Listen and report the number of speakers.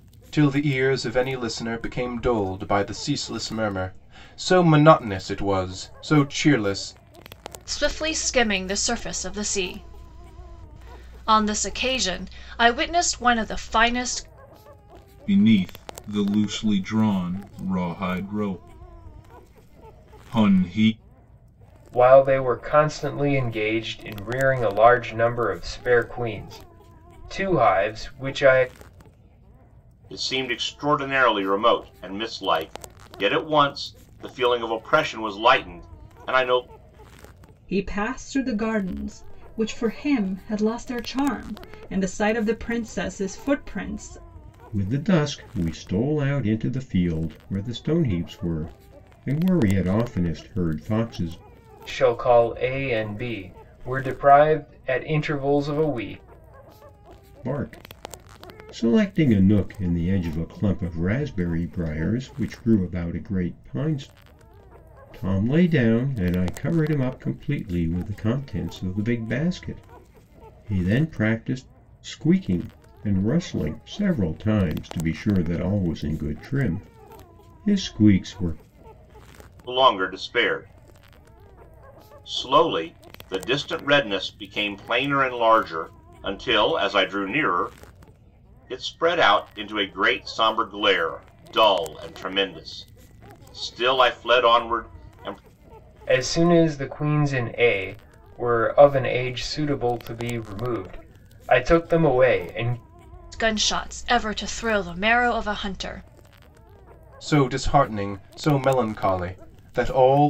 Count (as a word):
seven